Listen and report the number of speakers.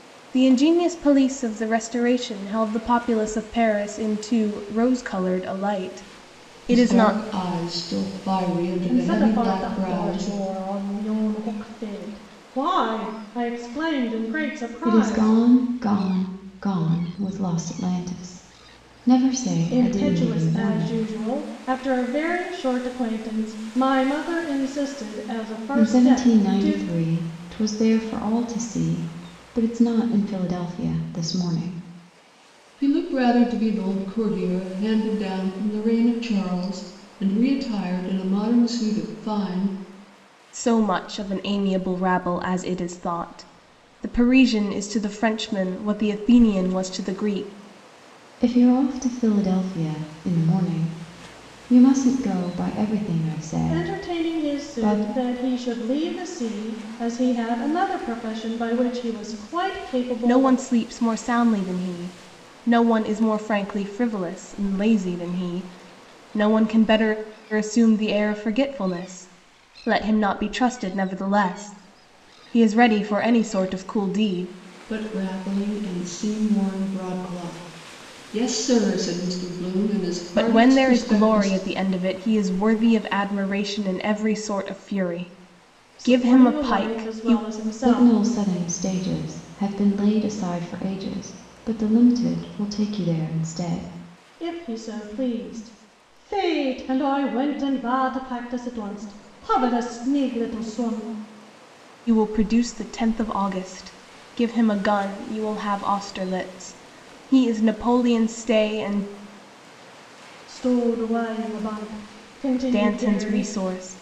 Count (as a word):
four